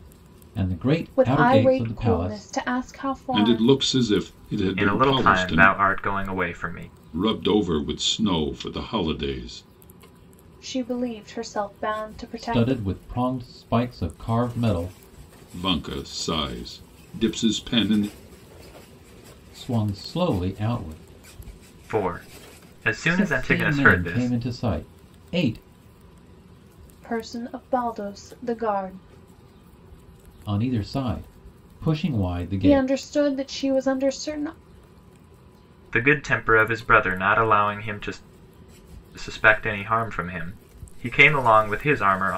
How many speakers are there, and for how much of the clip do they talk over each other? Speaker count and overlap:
four, about 12%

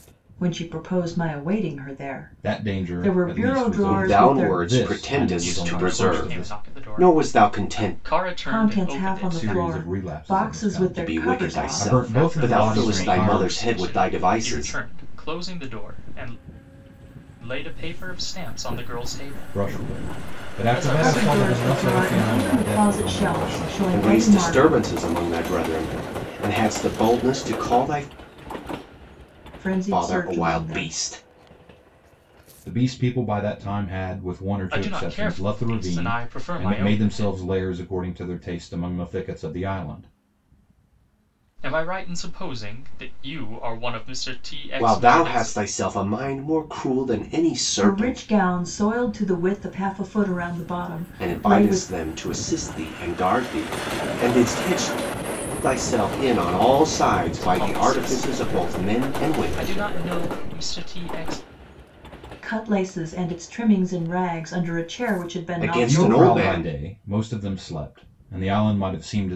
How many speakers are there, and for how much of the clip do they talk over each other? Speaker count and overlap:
four, about 39%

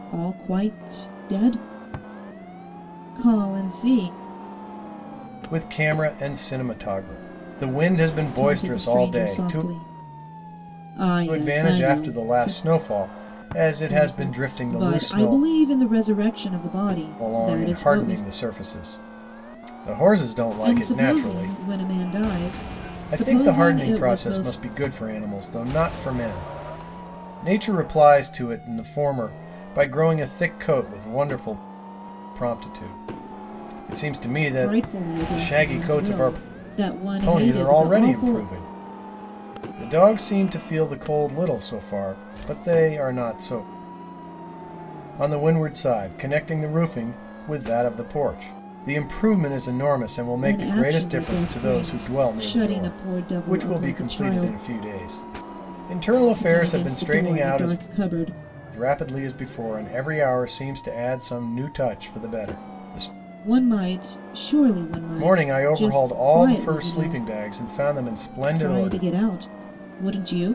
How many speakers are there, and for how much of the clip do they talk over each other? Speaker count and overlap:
two, about 27%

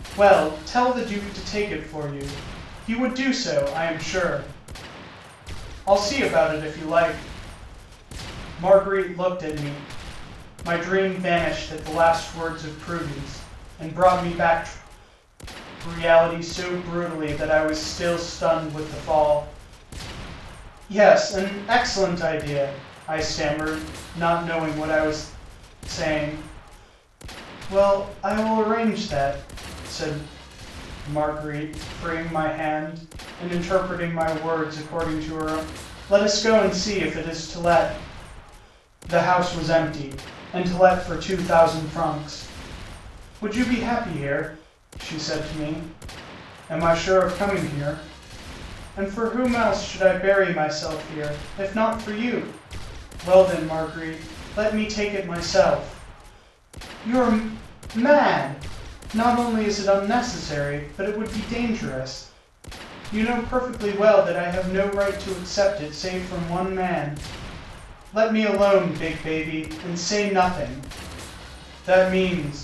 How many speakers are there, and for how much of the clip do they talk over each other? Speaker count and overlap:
one, no overlap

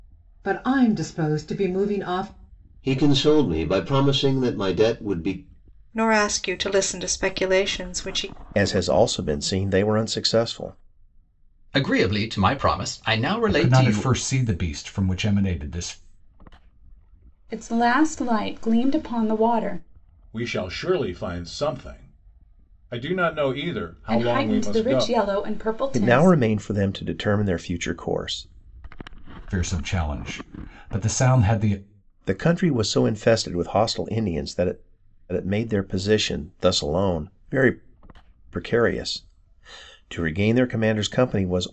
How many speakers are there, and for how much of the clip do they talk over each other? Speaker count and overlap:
eight, about 5%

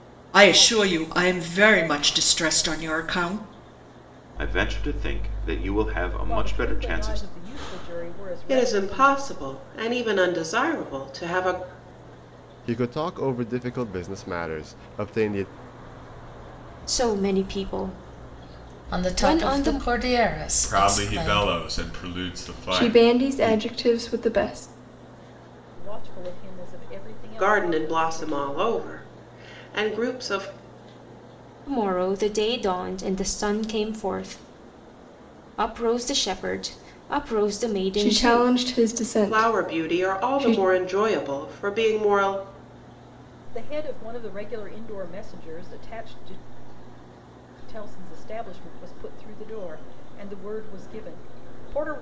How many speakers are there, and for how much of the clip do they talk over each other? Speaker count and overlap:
nine, about 15%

